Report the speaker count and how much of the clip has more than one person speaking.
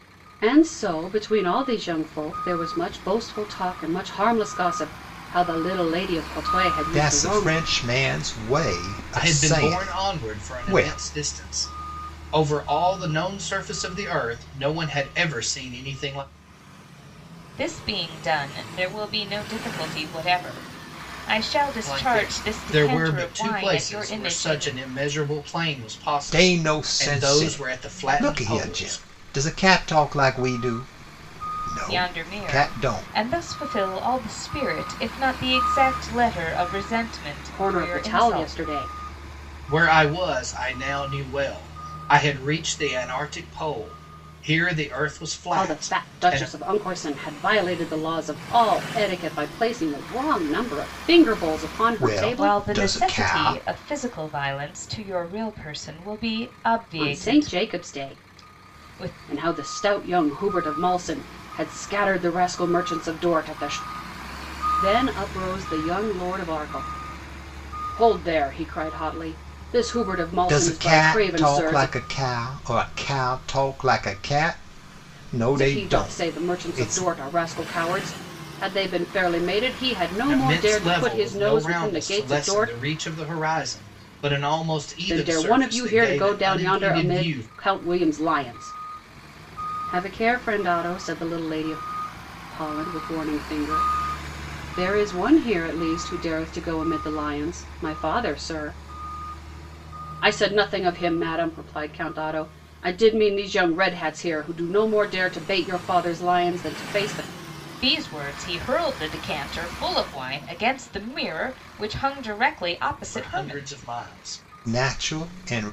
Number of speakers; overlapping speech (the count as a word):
four, about 21%